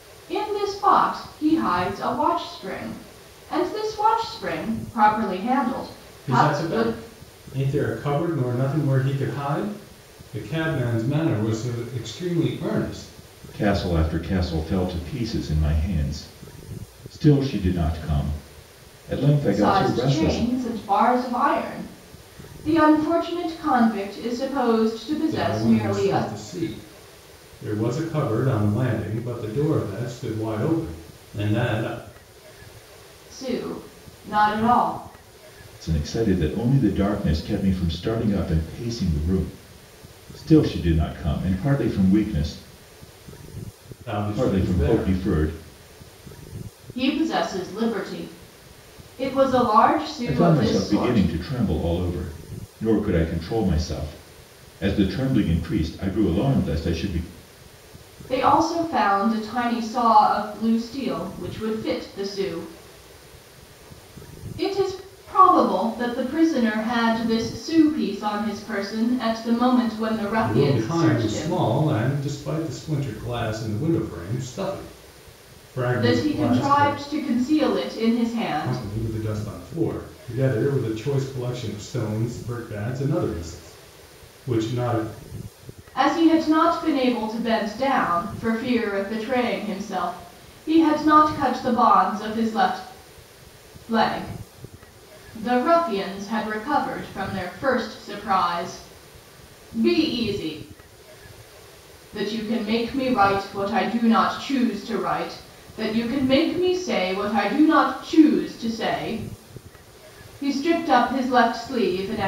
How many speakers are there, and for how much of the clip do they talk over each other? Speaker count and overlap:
3, about 7%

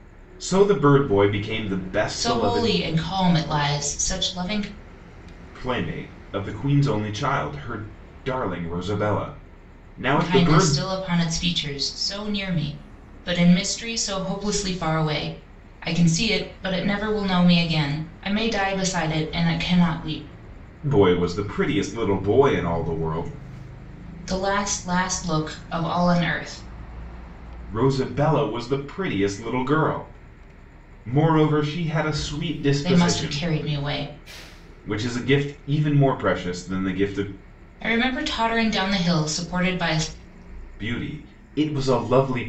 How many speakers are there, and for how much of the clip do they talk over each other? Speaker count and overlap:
2, about 4%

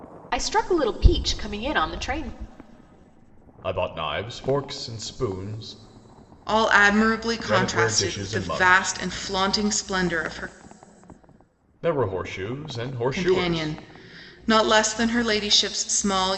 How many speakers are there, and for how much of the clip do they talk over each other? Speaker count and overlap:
3, about 14%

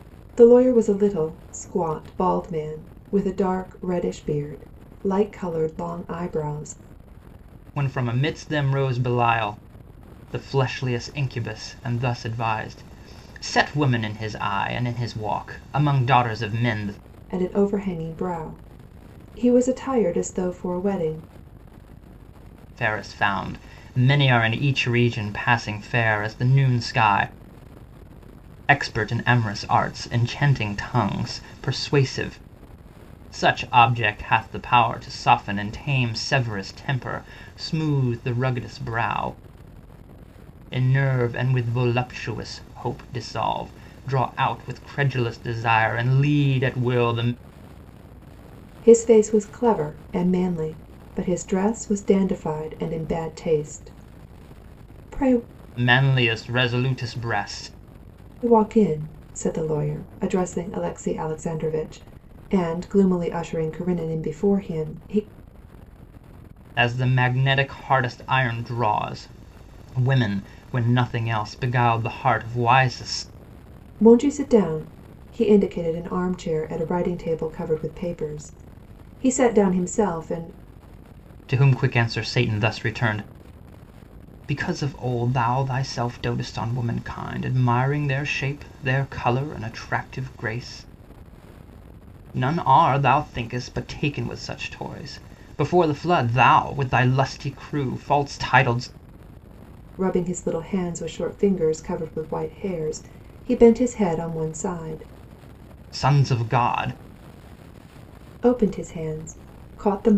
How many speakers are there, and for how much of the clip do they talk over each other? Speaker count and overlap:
2, no overlap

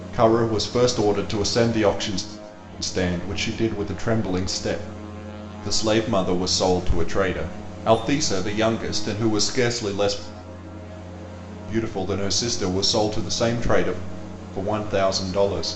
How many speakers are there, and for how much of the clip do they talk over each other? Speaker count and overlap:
1, no overlap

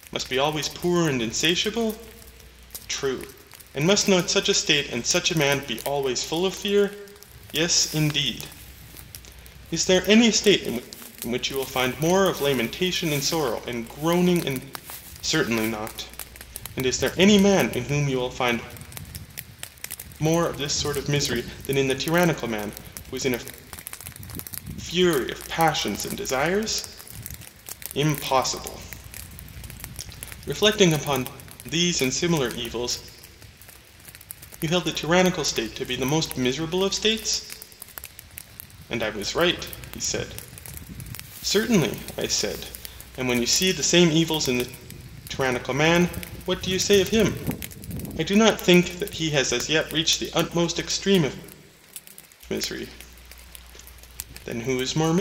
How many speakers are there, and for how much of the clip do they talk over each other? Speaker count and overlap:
1, no overlap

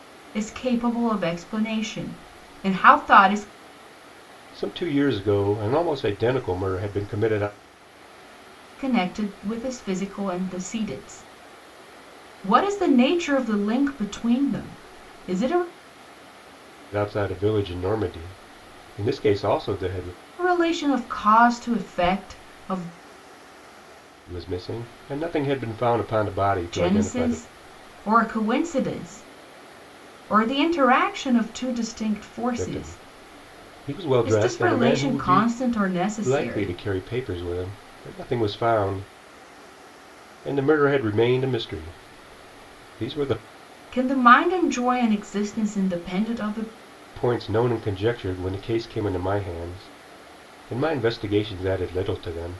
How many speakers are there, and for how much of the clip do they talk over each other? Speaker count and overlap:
2, about 6%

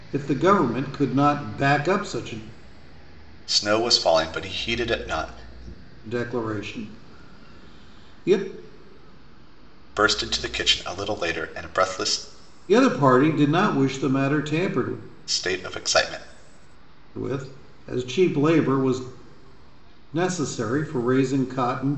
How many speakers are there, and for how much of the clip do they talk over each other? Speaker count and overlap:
2, no overlap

